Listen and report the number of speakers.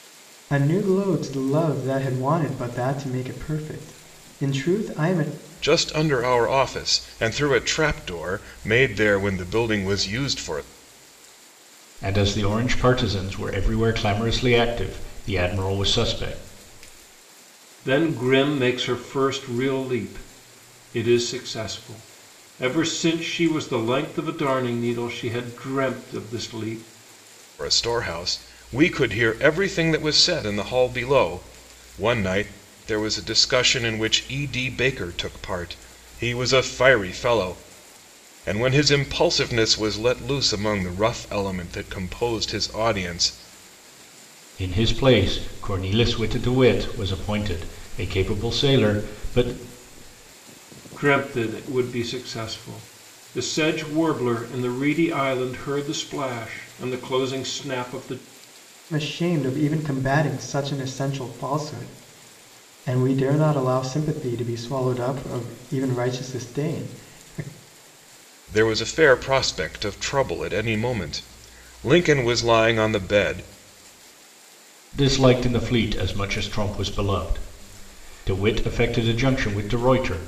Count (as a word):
four